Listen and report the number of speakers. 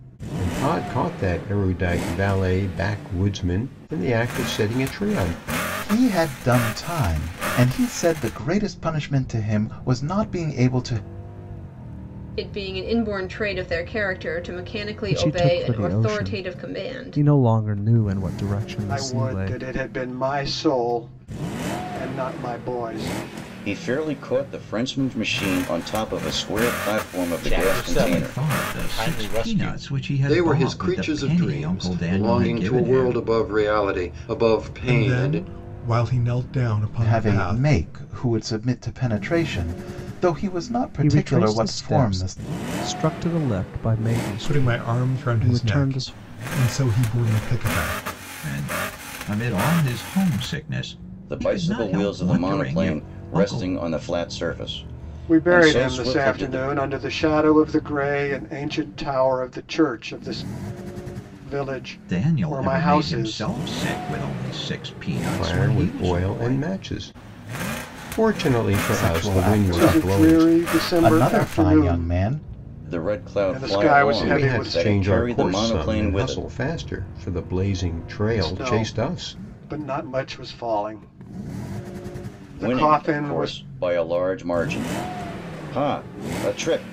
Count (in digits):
10